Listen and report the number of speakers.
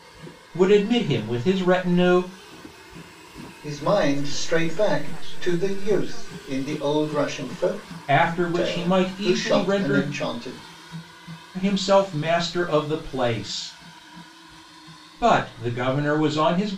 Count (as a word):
three